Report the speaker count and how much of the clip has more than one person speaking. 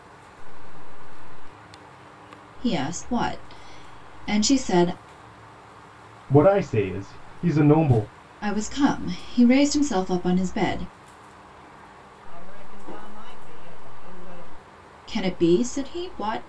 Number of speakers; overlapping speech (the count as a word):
three, no overlap